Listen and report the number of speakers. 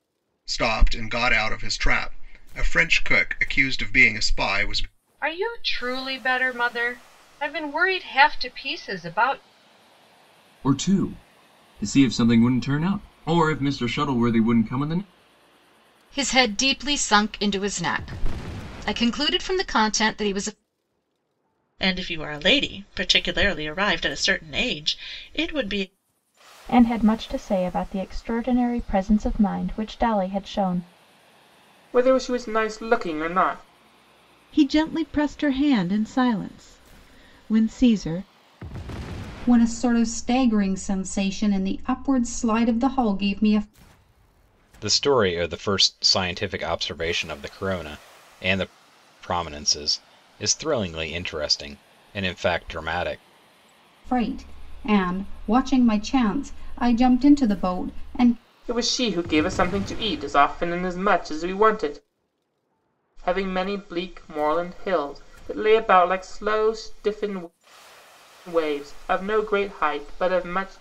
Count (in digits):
10